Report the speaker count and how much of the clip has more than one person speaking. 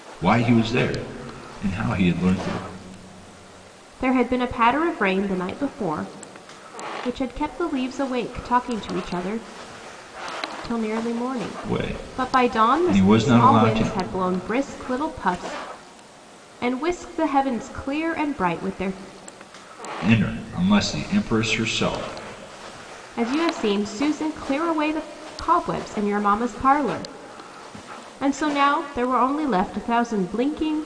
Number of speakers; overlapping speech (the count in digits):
2, about 7%